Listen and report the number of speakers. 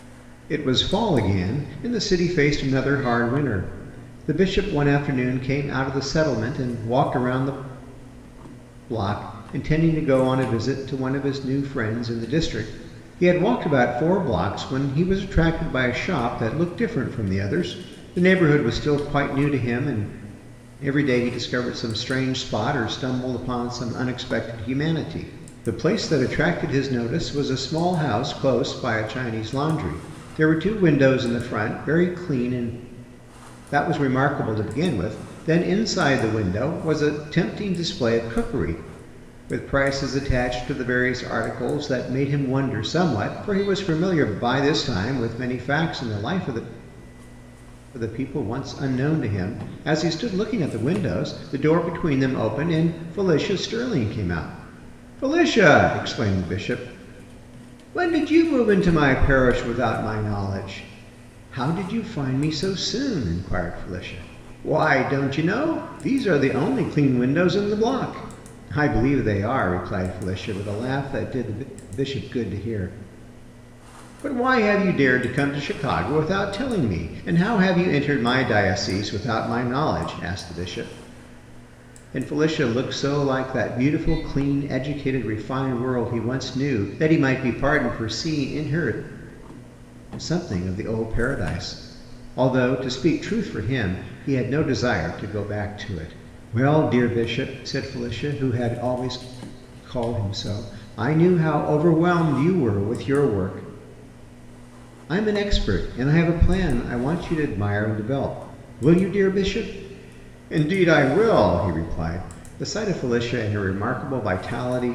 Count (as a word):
one